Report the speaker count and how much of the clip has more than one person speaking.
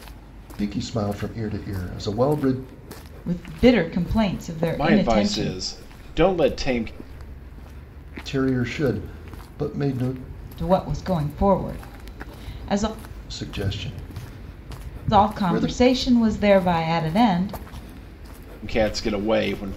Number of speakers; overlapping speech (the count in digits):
3, about 7%